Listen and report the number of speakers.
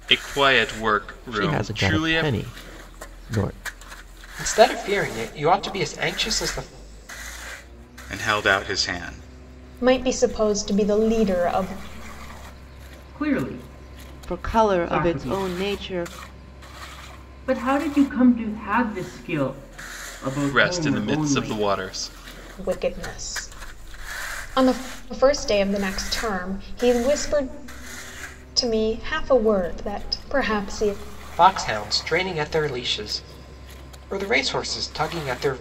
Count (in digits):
7